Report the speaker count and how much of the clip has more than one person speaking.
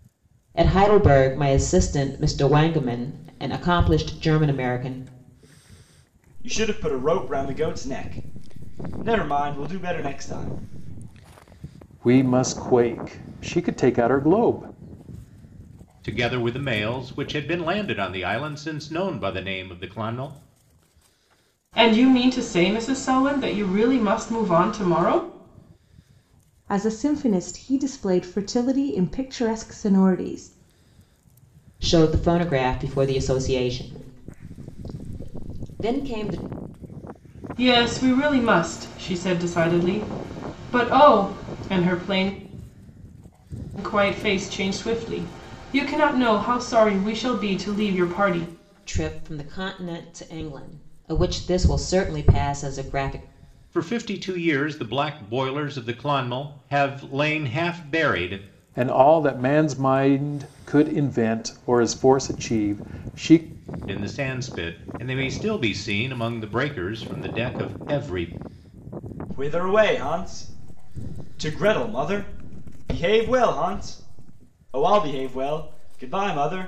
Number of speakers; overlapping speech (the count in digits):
6, no overlap